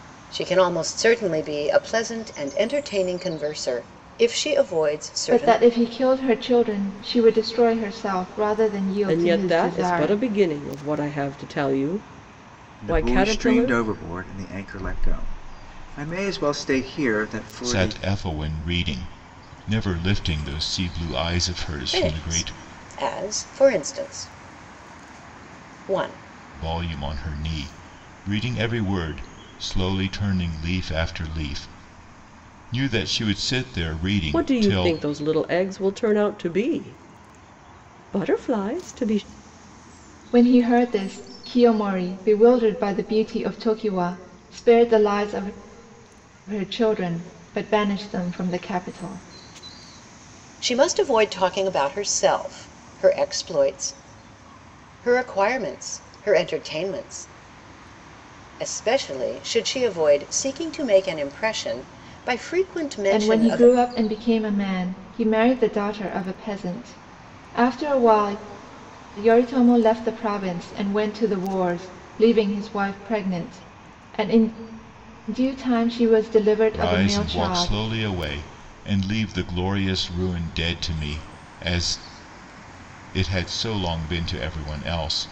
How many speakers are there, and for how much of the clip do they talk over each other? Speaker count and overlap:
5, about 7%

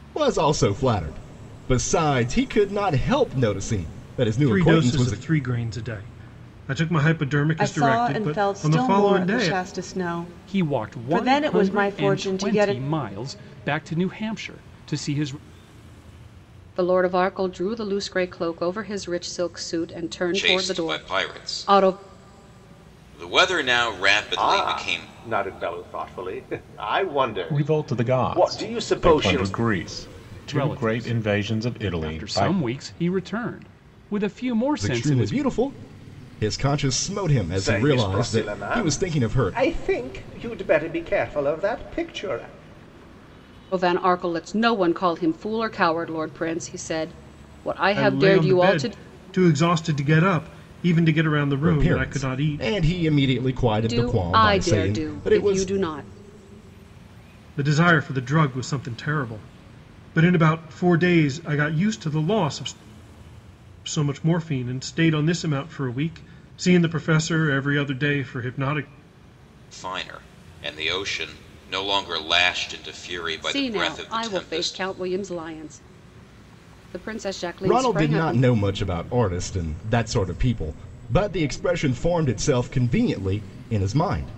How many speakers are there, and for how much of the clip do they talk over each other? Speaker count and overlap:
8, about 24%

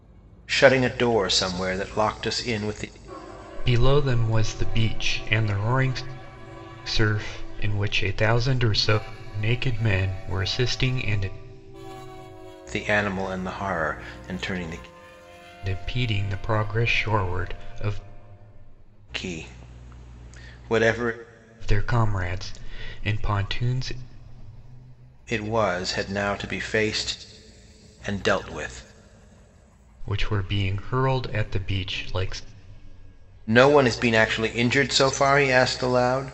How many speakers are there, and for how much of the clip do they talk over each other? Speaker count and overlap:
2, no overlap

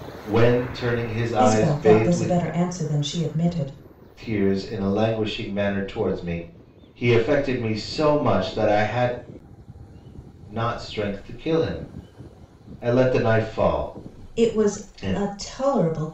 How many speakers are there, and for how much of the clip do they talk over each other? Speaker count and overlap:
2, about 12%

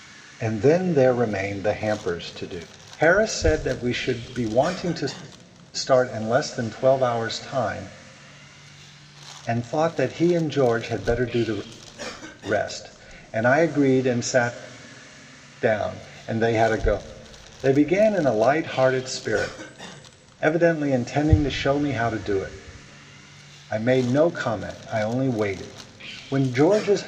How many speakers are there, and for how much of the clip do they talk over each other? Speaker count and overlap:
1, no overlap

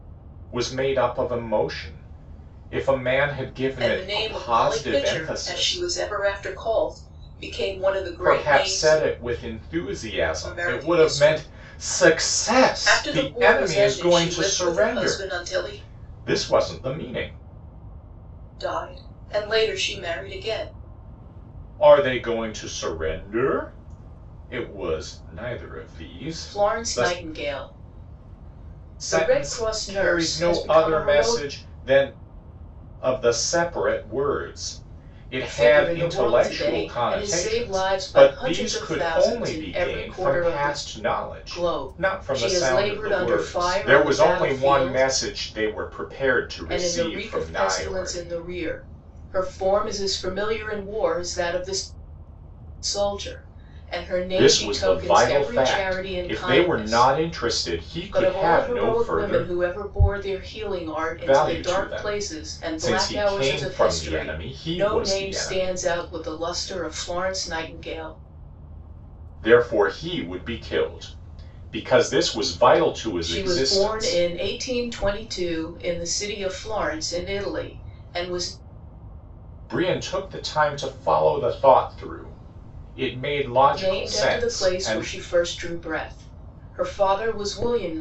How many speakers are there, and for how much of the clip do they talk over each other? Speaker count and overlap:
2, about 38%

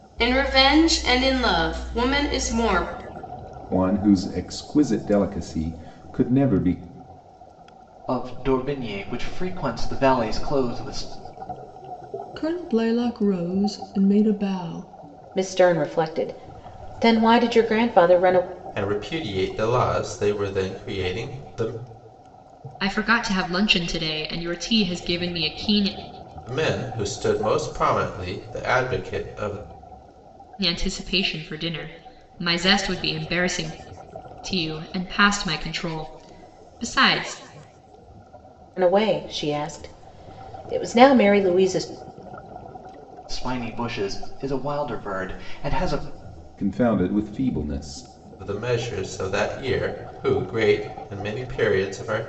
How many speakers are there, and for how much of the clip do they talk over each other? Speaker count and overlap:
7, no overlap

